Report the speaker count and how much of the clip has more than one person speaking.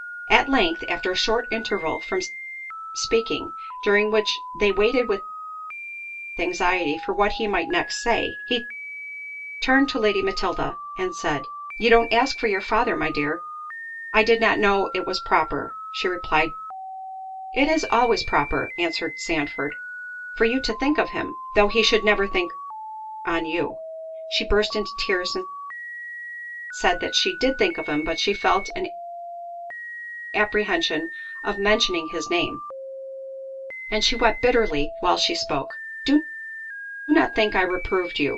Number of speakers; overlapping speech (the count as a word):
one, no overlap